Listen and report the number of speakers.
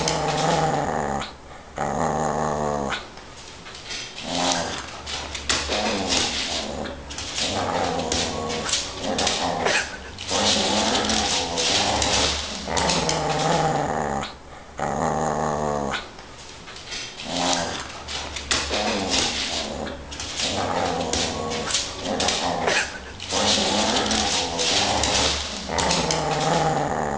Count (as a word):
zero